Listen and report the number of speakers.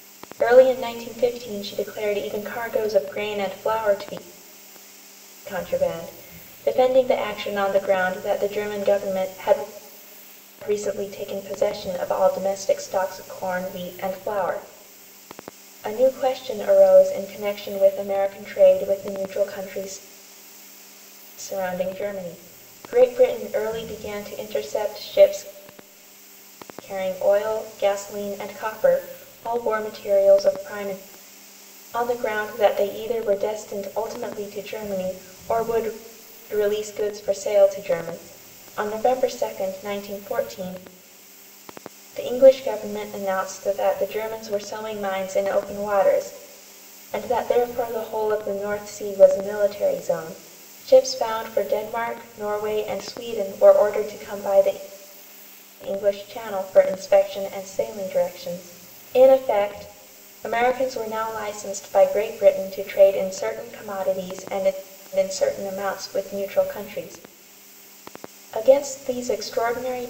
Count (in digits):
1